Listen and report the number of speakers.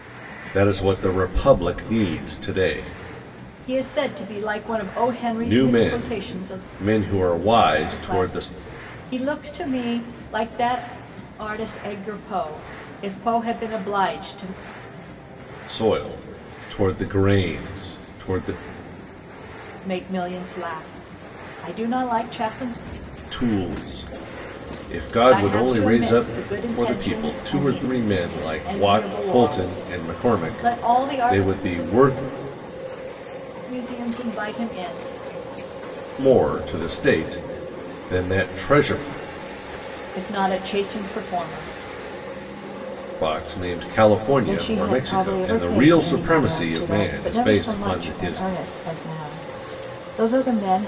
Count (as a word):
two